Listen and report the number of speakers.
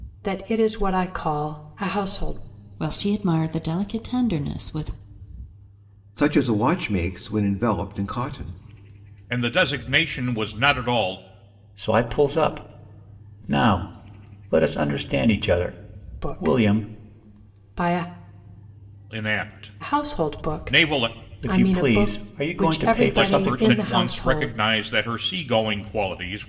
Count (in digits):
5